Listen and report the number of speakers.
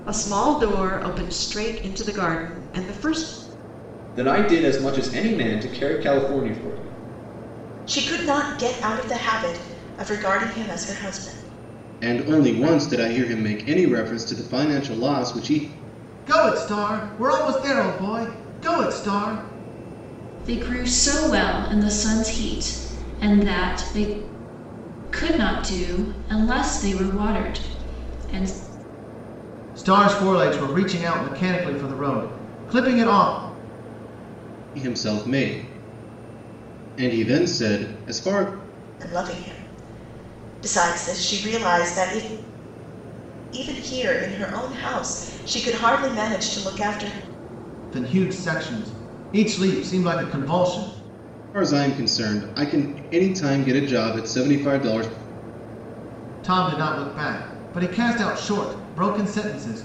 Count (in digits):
6